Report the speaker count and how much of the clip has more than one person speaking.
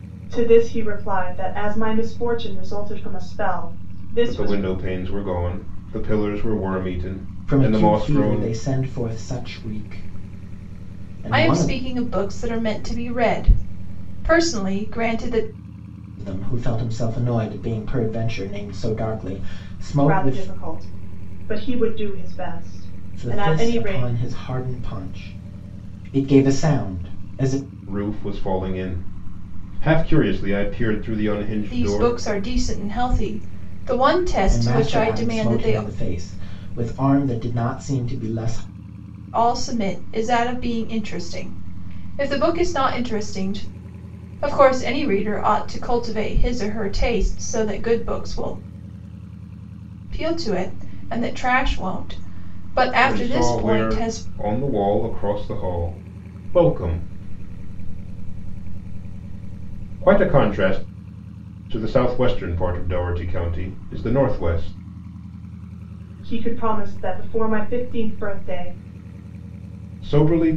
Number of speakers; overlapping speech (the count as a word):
four, about 9%